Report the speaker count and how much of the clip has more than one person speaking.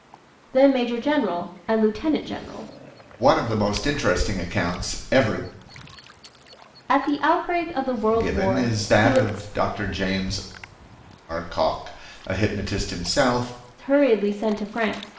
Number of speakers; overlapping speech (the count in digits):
2, about 8%